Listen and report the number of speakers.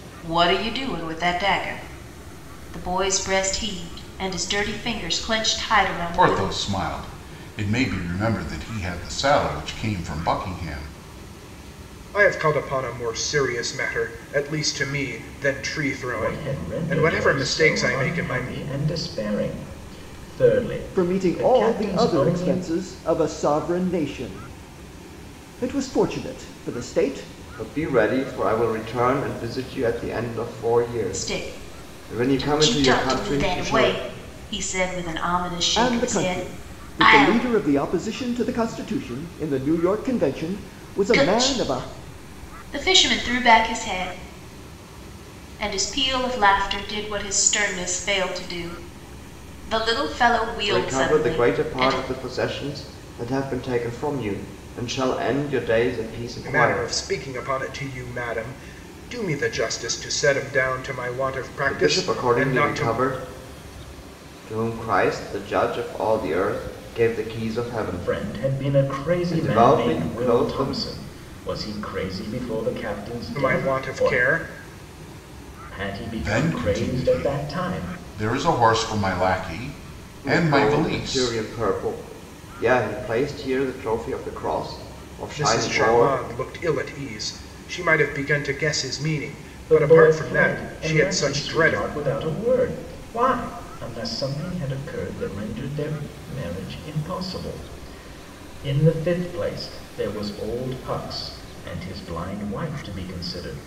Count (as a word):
six